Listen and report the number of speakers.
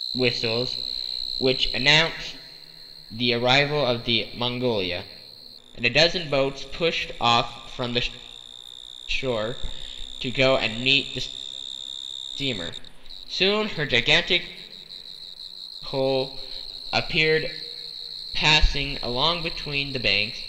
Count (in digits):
1